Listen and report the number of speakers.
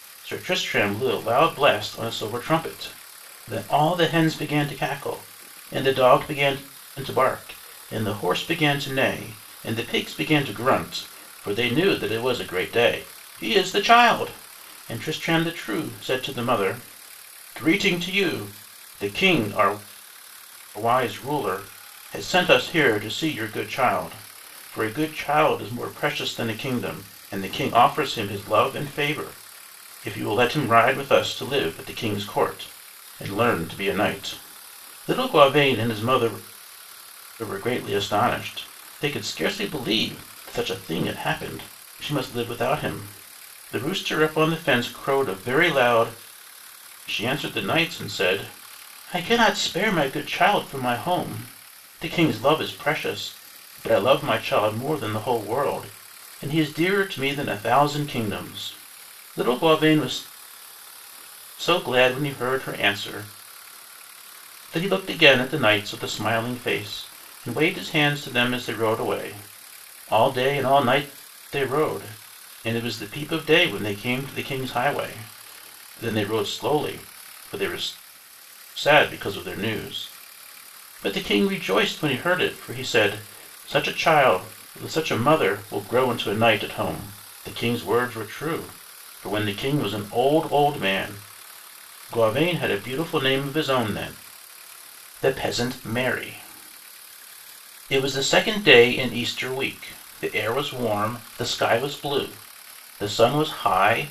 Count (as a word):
one